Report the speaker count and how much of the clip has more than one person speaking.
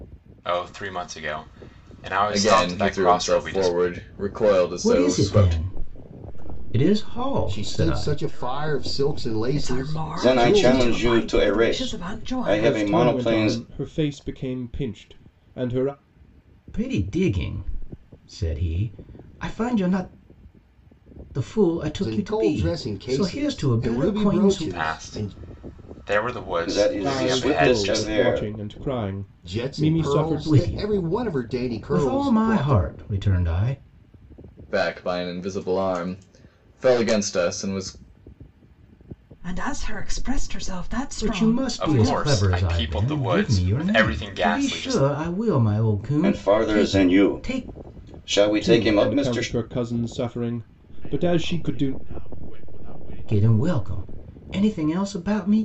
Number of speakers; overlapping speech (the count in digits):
8, about 48%